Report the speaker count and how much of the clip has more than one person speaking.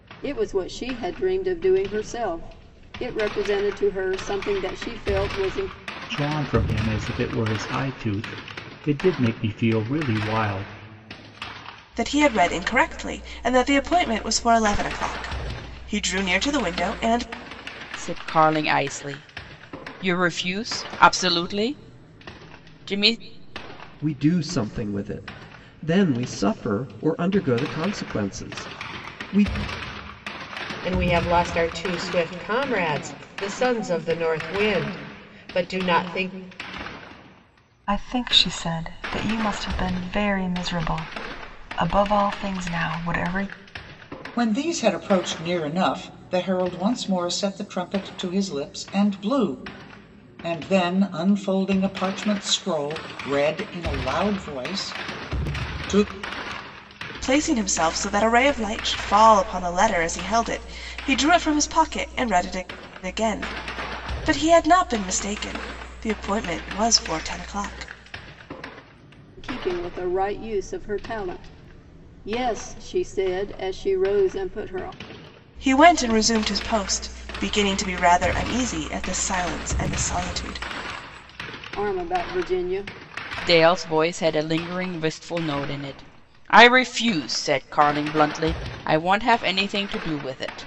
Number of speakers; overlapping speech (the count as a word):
eight, no overlap